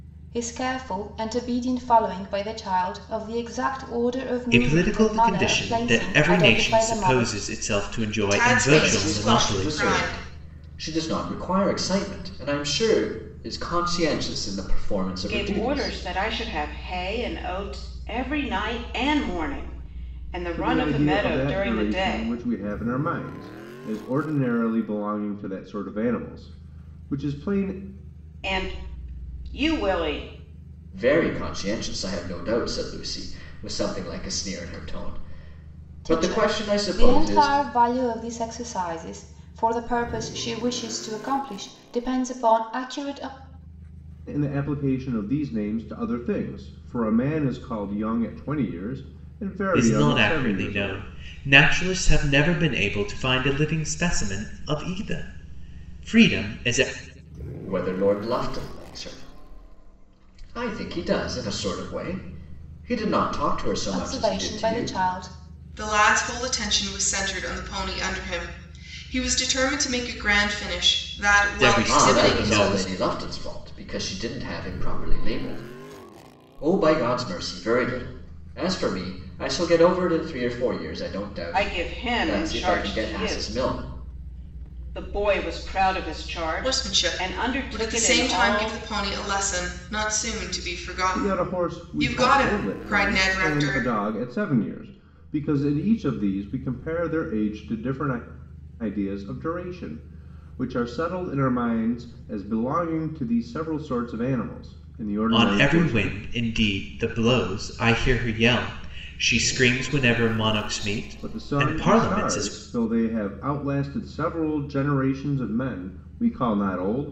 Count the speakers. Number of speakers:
six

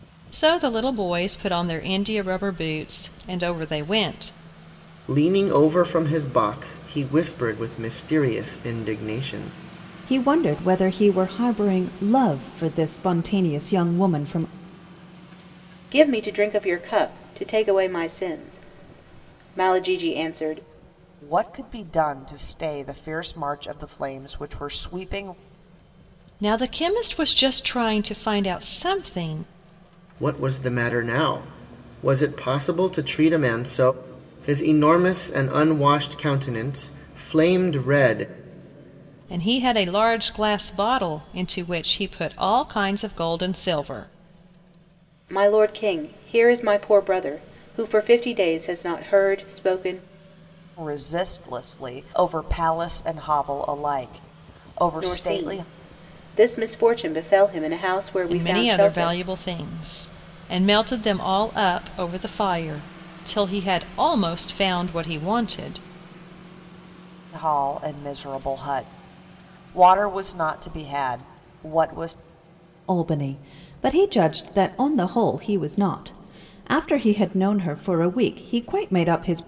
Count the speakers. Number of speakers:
five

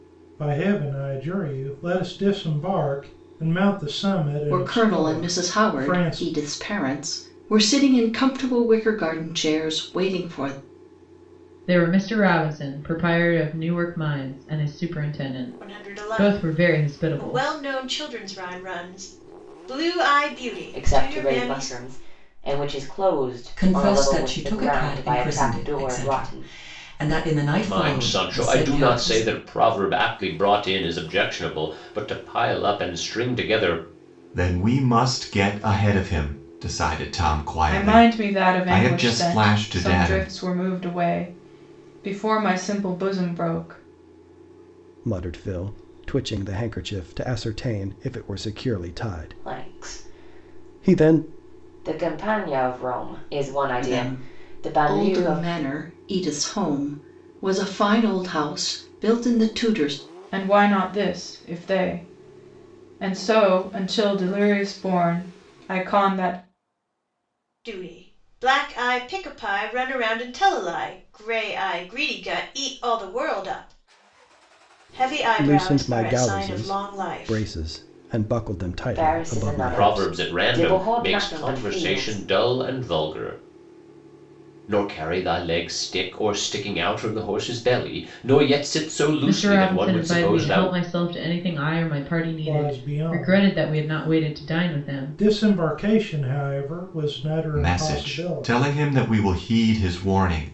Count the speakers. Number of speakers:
ten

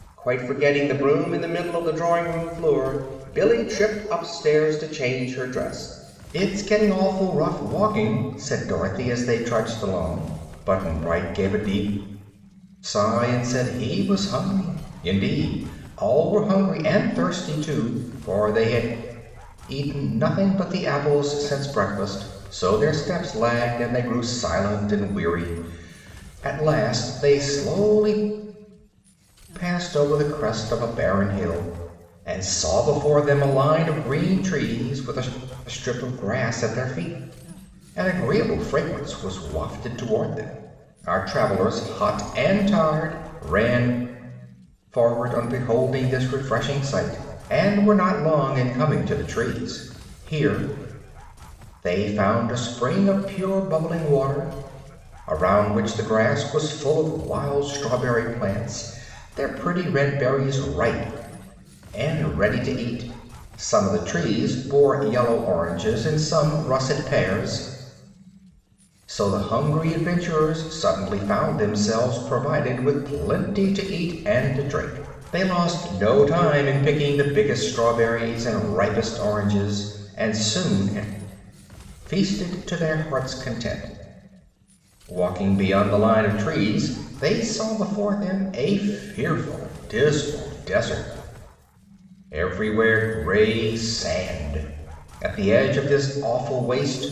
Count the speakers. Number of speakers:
one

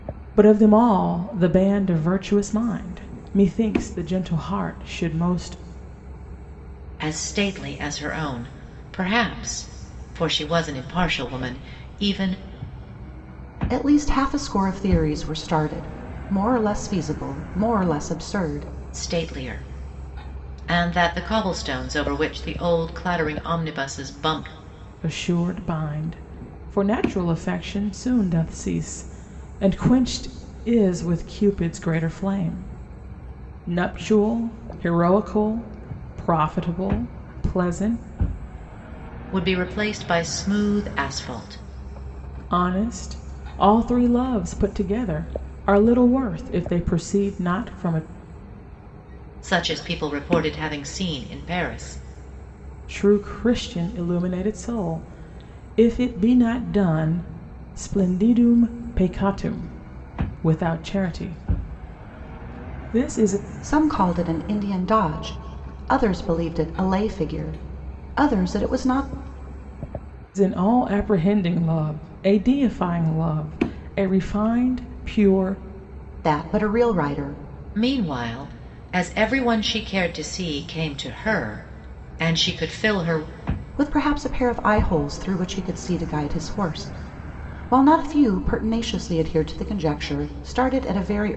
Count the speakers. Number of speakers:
three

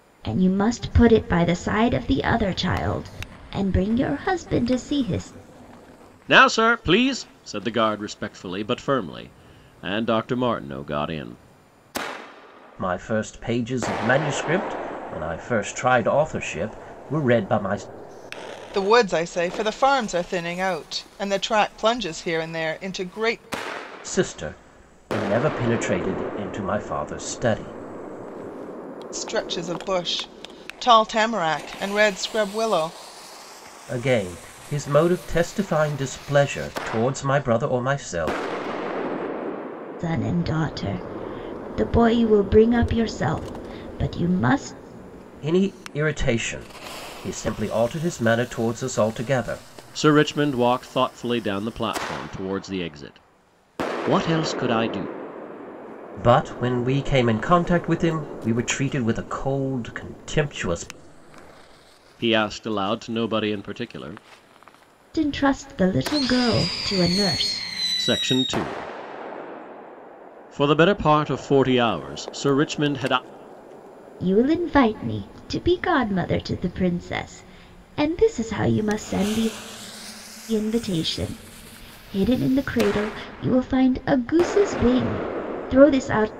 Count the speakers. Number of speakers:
four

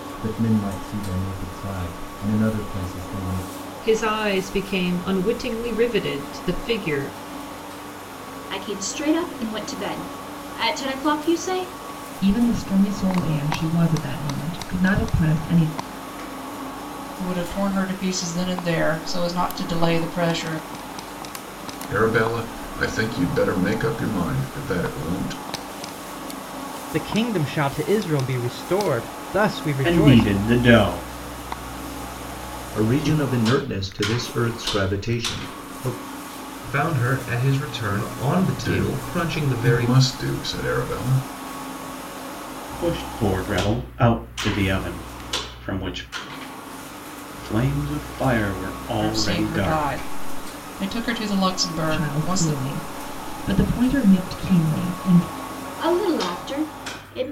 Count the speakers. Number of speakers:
ten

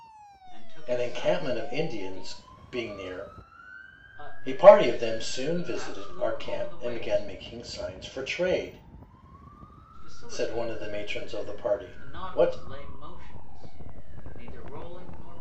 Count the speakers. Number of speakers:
two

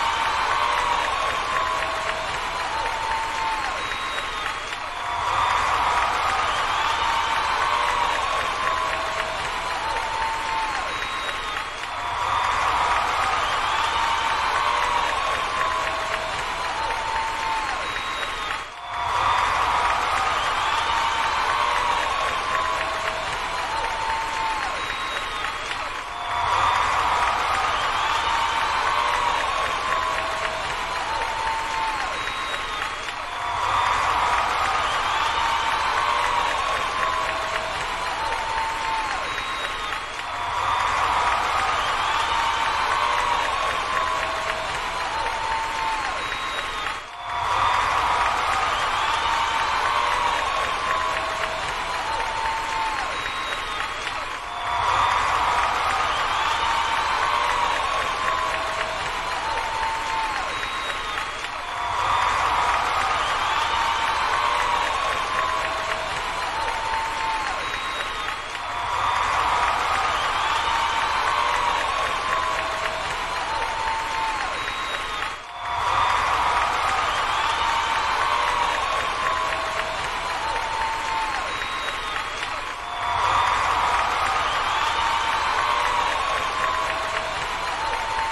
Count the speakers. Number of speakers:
zero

